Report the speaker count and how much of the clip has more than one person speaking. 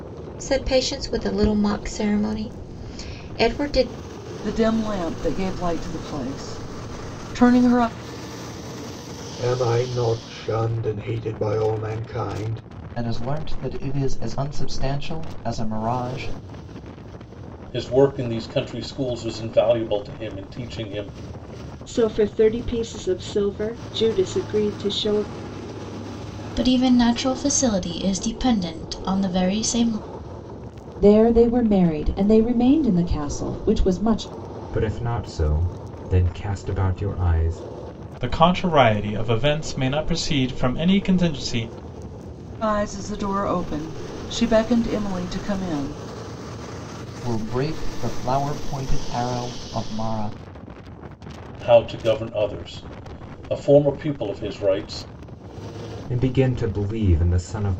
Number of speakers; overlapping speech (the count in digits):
10, no overlap